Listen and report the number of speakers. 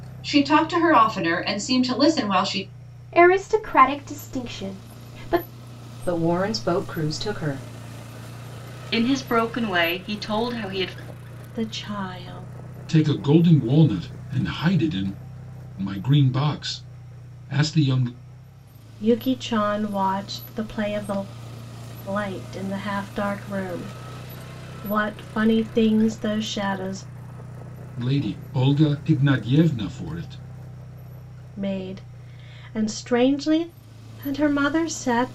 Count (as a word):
six